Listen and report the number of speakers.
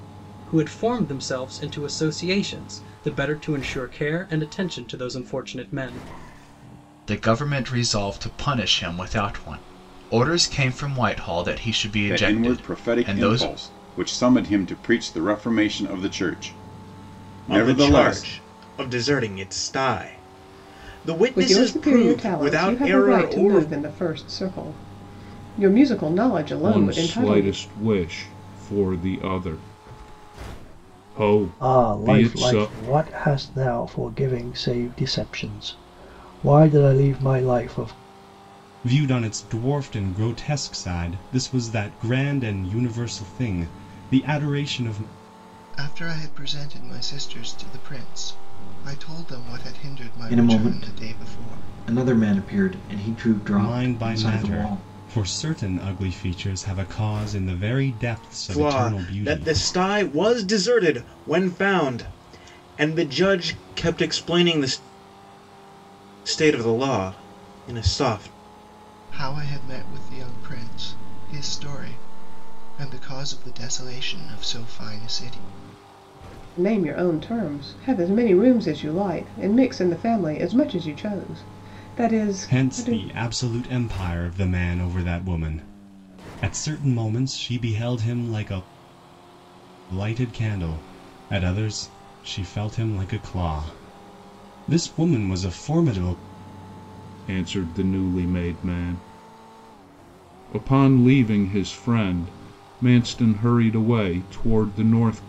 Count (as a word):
ten